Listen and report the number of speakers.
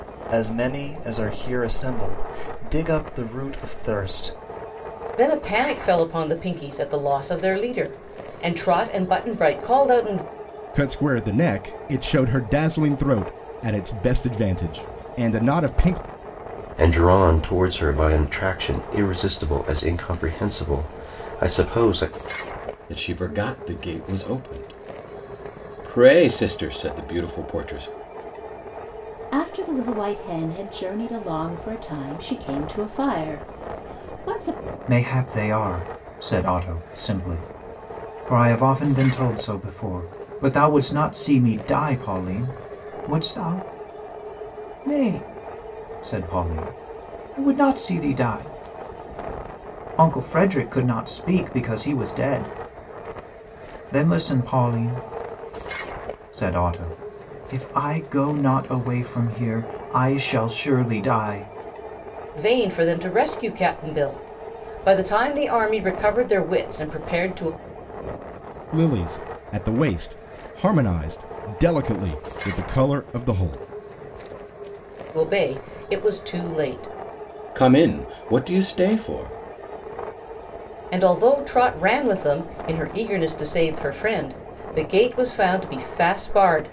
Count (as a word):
seven